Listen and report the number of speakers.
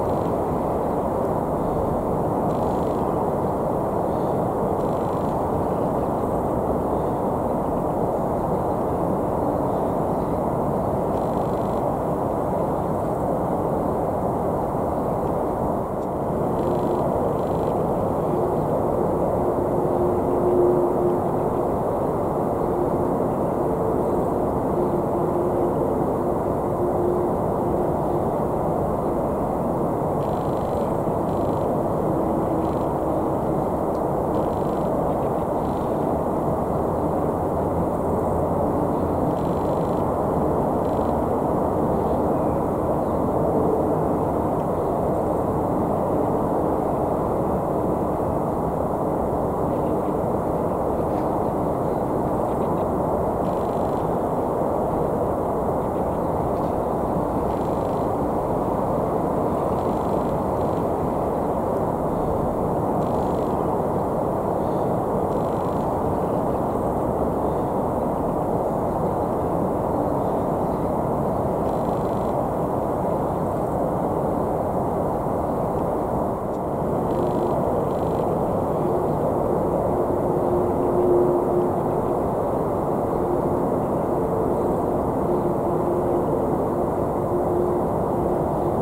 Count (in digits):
0